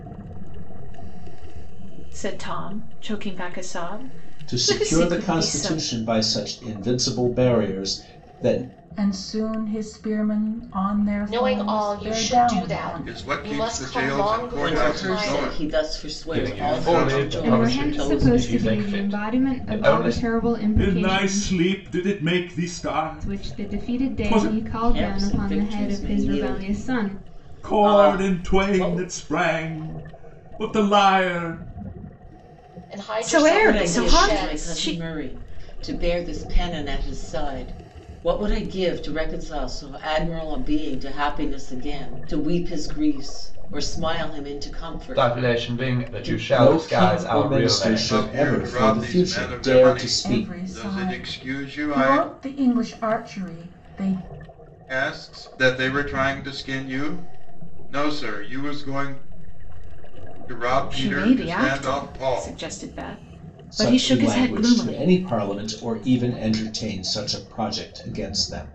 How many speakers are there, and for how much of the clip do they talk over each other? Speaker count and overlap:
ten, about 54%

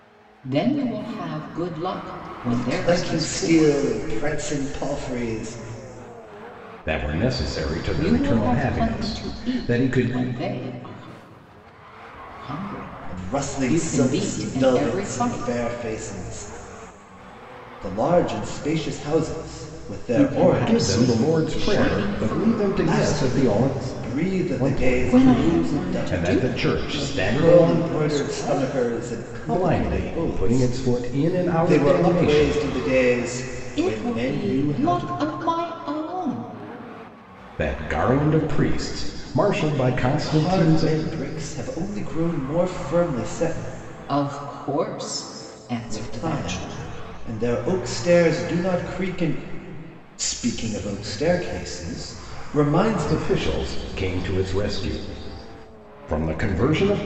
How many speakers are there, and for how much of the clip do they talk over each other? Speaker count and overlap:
three, about 36%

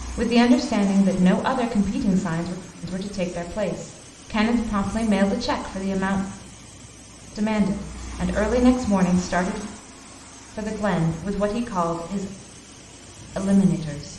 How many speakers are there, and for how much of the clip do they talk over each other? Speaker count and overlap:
one, no overlap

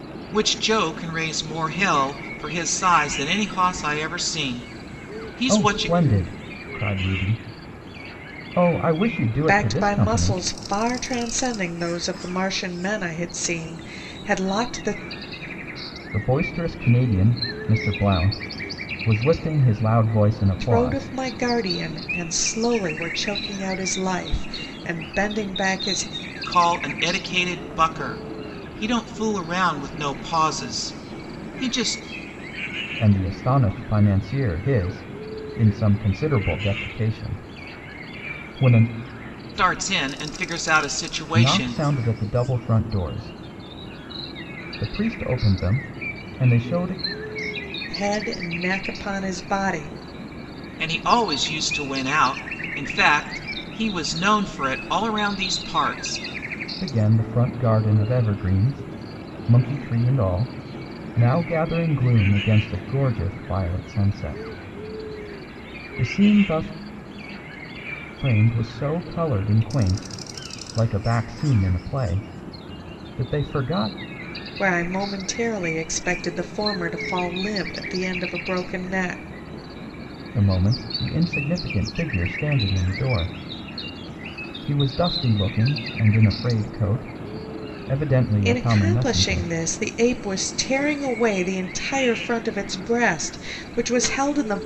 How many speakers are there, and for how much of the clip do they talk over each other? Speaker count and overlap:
three, about 4%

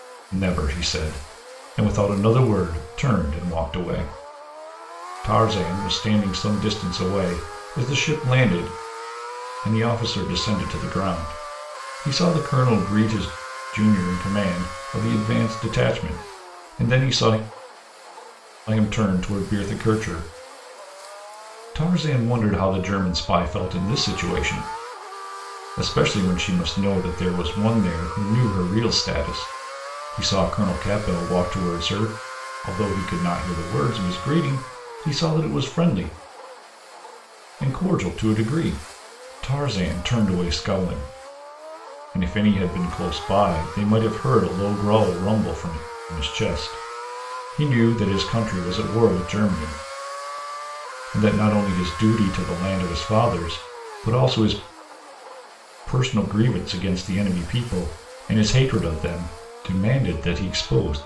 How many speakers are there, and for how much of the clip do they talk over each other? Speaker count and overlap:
one, no overlap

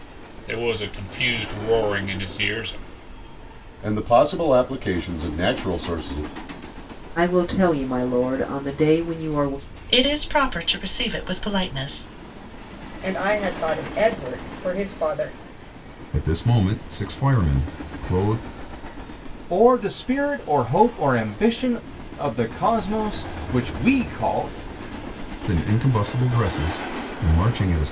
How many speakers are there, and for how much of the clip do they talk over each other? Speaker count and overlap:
seven, no overlap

